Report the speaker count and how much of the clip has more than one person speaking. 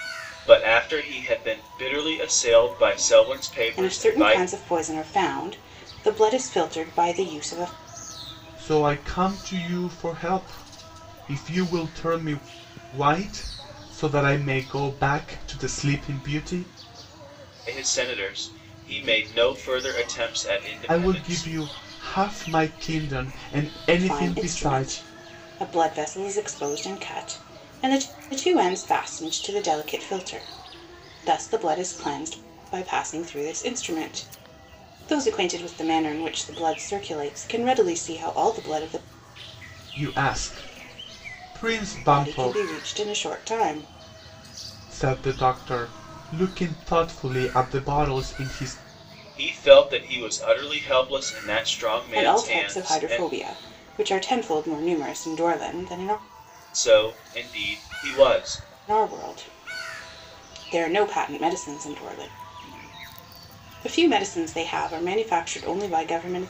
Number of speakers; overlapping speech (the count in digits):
3, about 6%